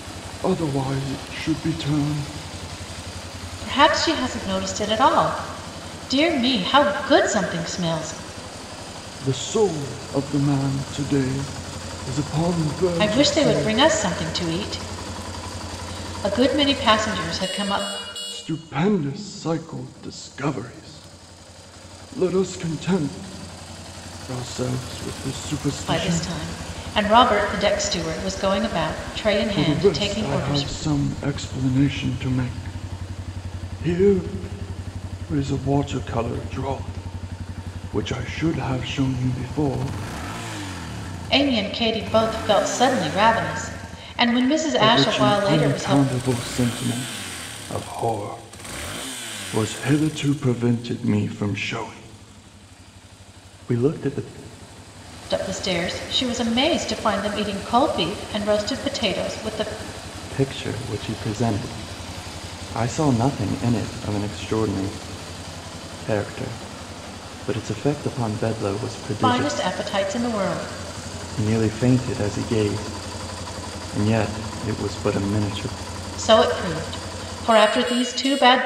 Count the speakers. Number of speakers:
two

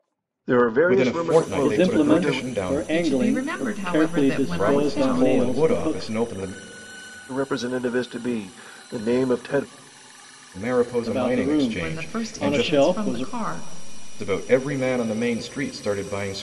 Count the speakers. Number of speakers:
four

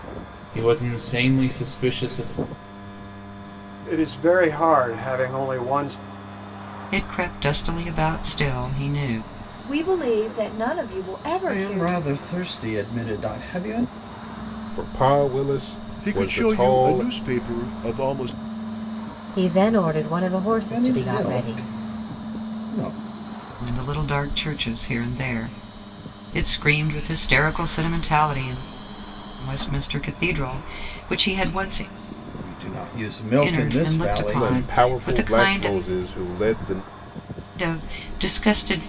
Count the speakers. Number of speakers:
eight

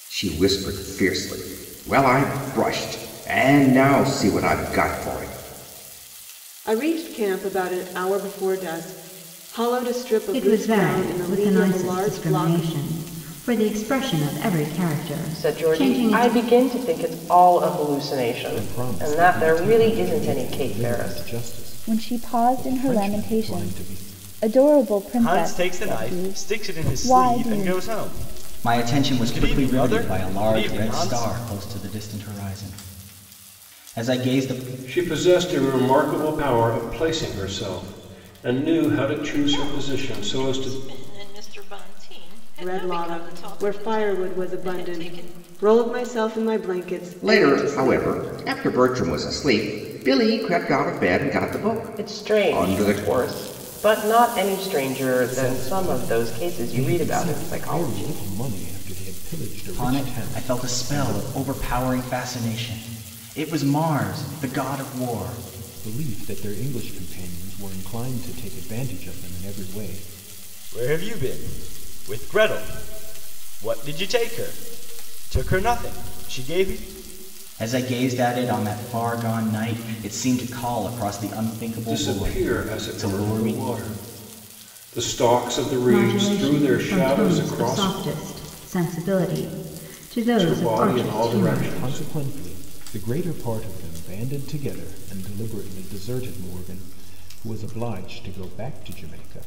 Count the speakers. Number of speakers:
ten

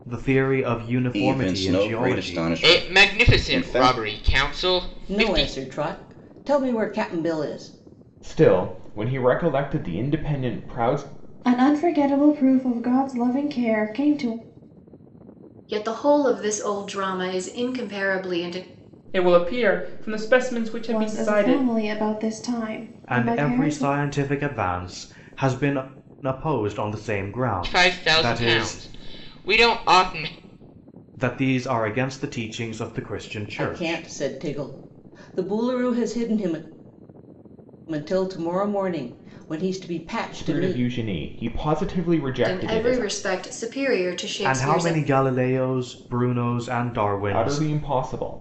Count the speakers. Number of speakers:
eight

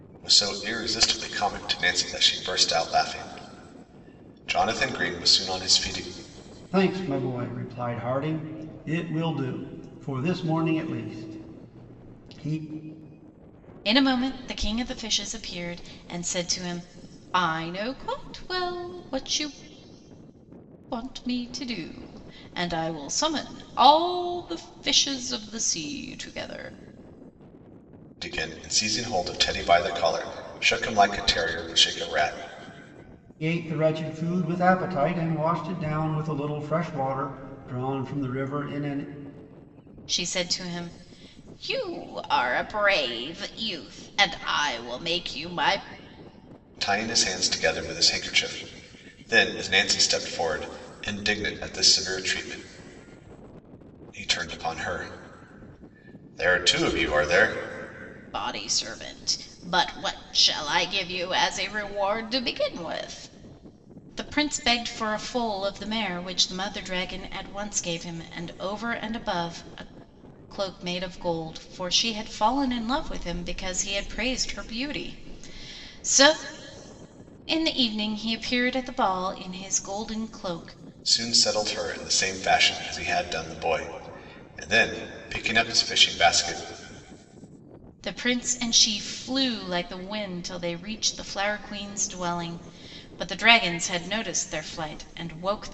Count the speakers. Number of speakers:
three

